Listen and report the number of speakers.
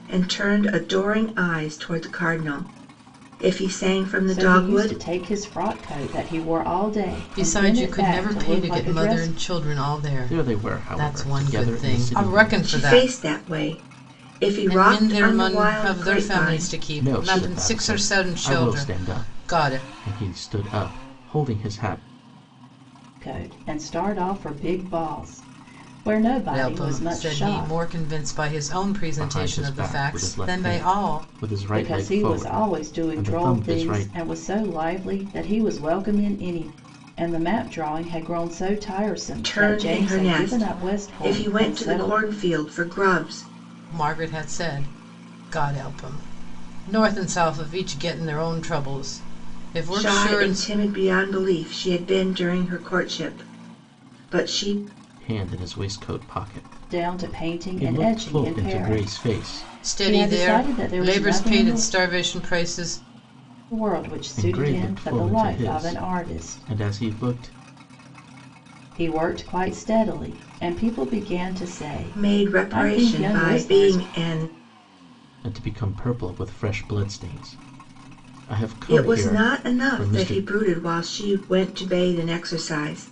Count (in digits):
4